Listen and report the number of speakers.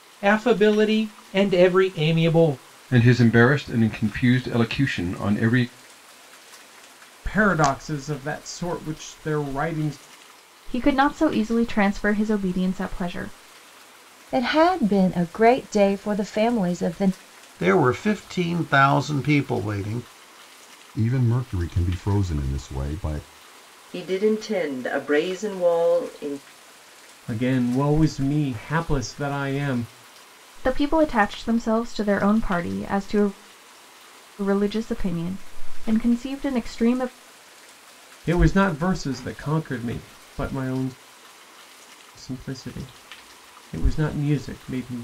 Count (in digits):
8